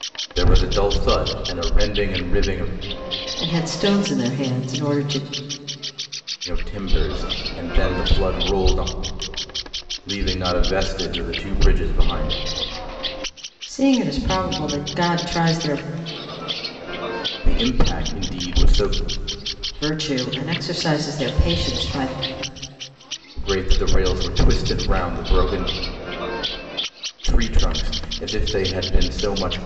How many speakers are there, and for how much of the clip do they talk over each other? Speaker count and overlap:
two, no overlap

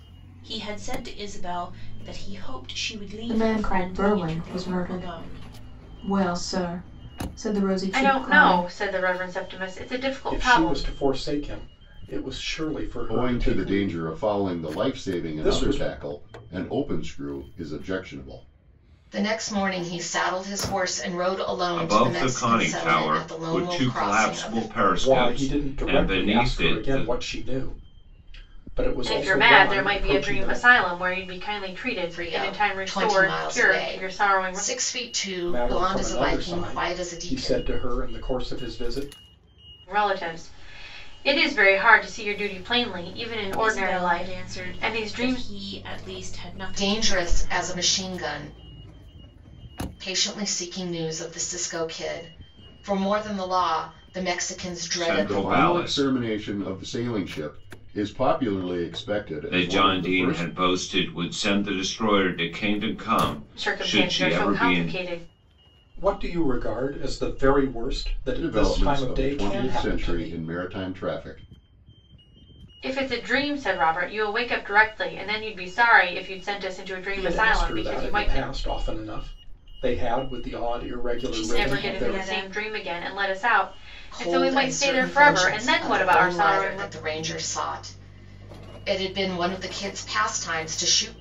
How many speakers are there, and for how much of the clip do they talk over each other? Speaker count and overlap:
seven, about 35%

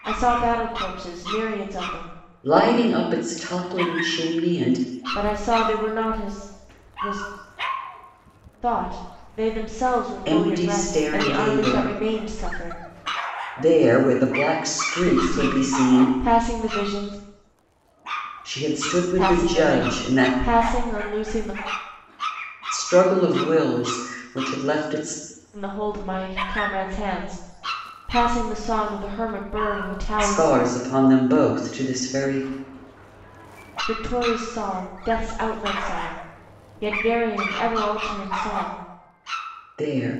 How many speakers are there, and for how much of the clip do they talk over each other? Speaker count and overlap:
two, about 11%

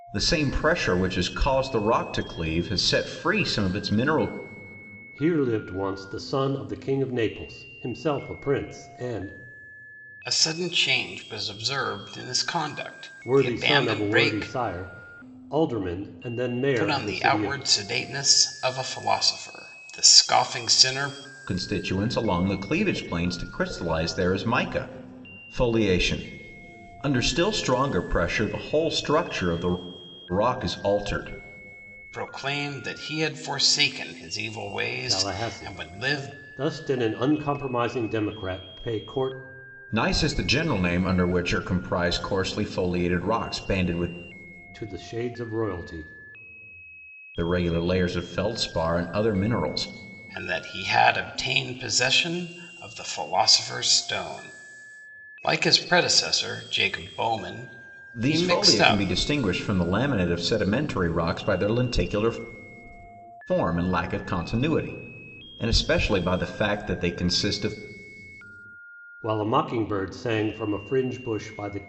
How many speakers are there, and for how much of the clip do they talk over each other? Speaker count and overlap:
three, about 6%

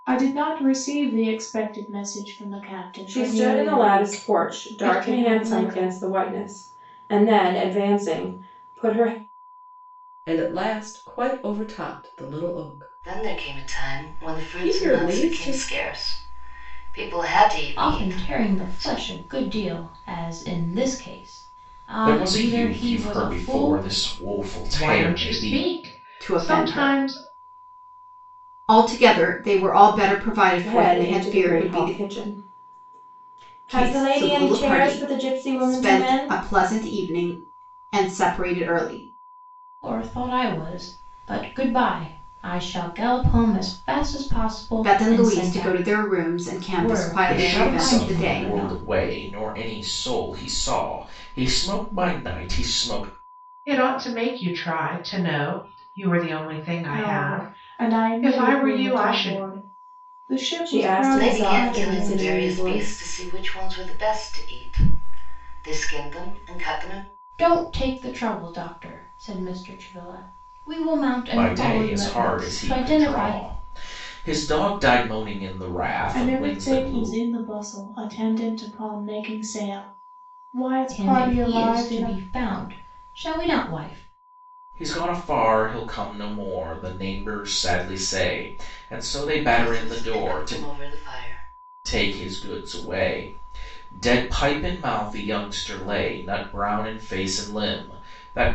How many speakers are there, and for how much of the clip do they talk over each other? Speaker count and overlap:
eight, about 29%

